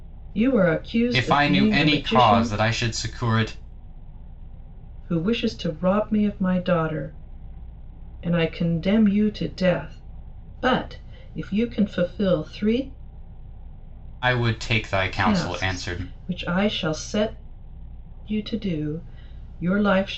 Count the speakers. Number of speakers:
two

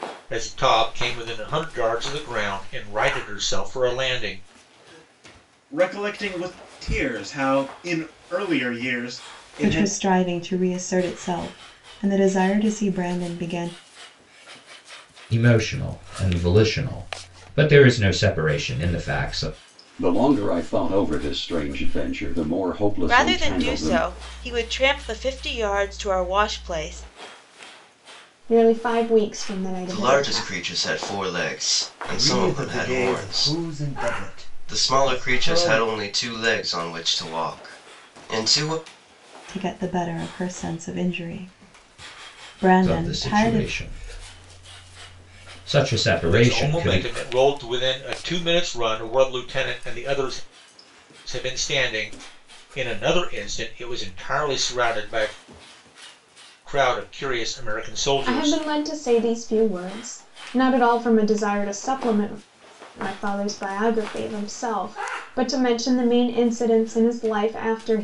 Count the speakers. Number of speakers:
nine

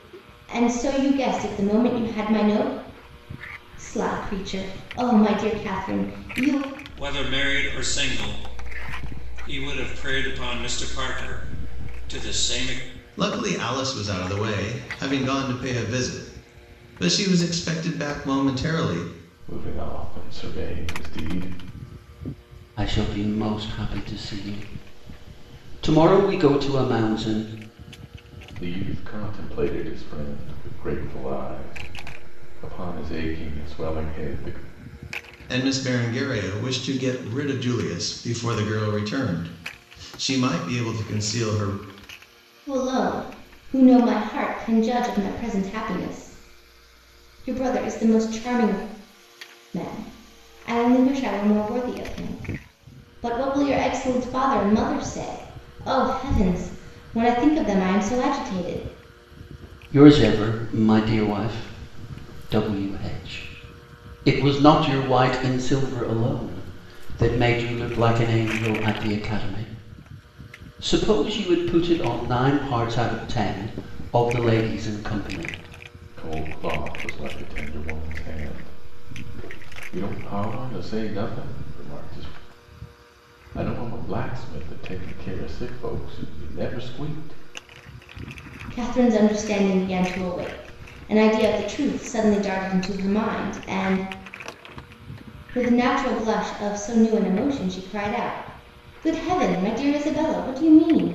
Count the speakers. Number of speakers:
five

